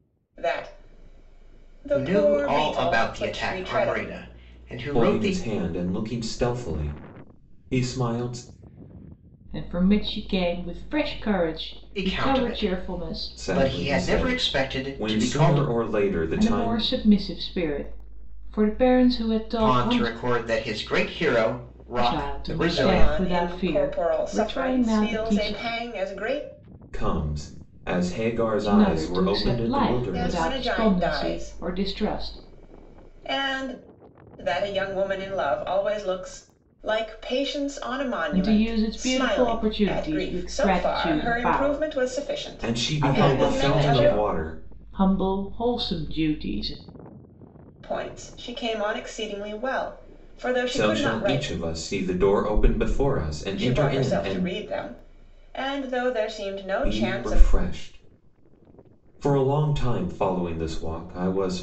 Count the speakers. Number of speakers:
4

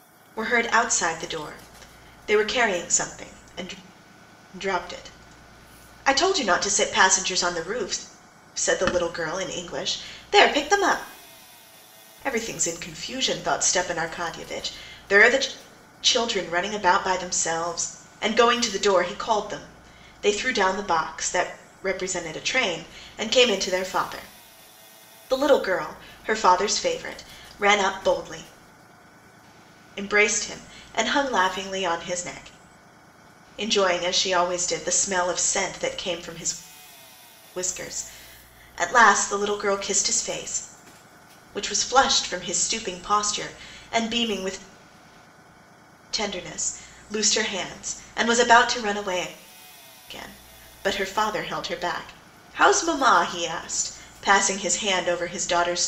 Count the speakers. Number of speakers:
1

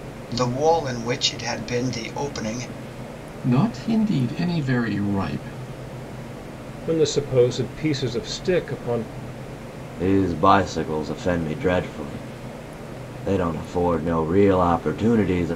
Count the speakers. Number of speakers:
4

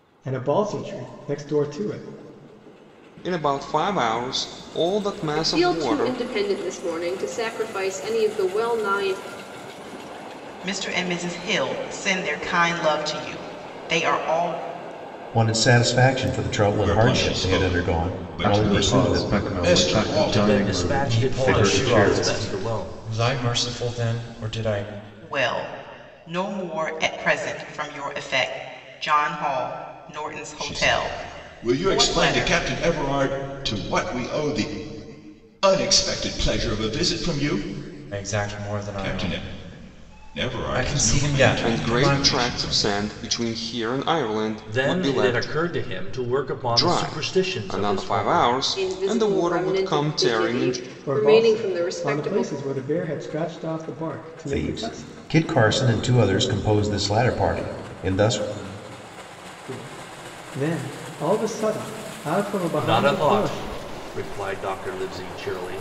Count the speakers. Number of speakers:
9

